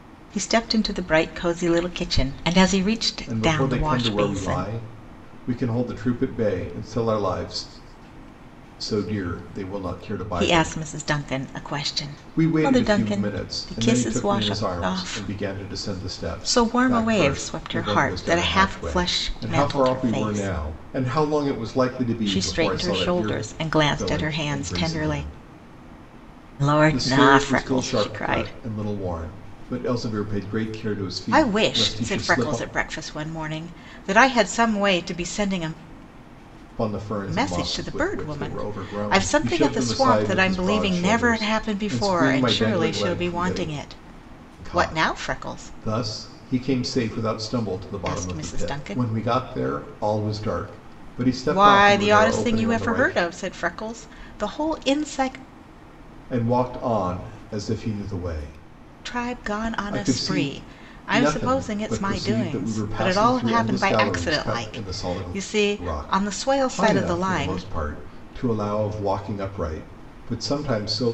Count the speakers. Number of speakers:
2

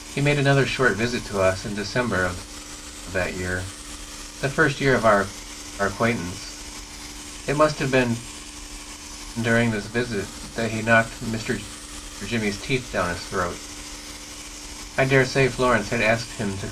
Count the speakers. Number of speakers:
1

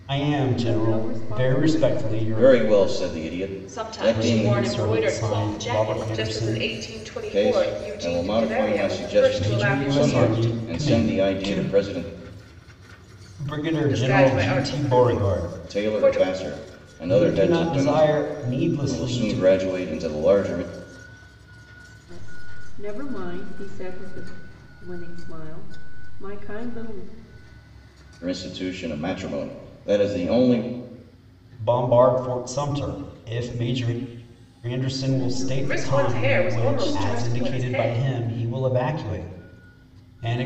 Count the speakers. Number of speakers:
4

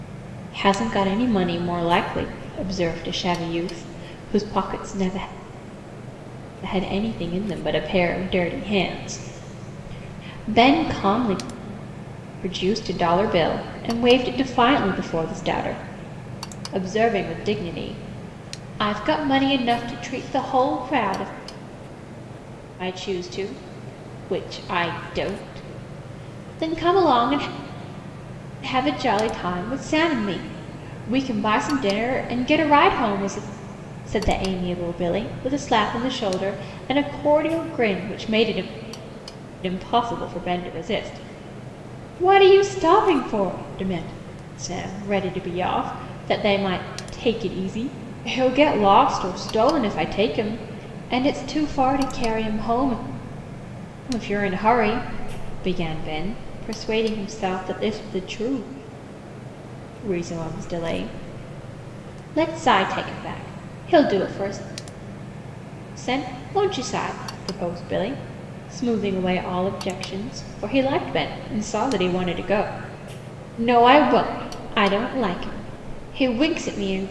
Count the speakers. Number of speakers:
1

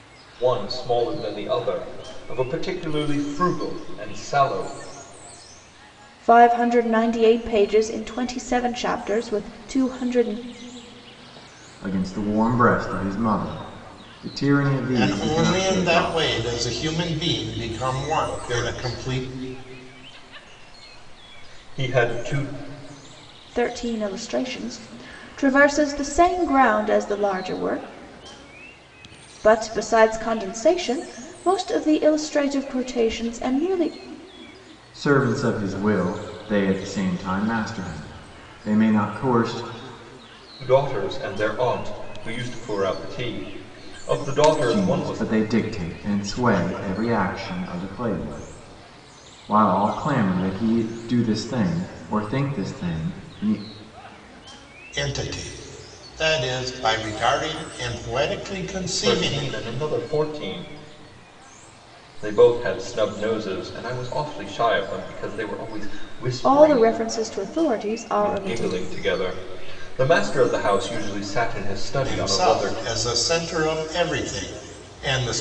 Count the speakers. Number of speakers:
4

